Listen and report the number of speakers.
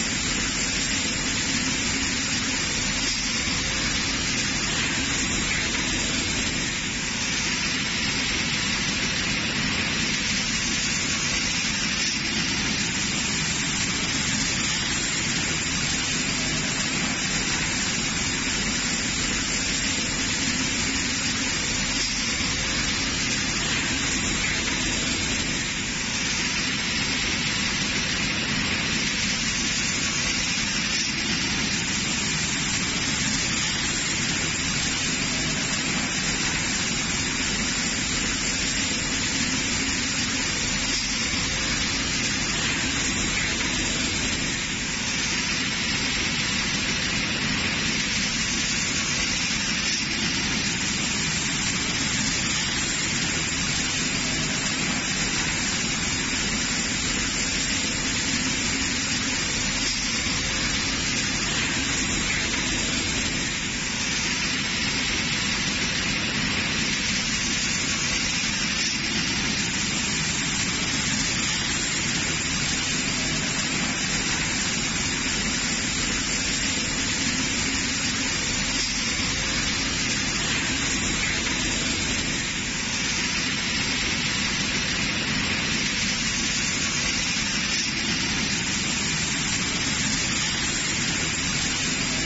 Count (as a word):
zero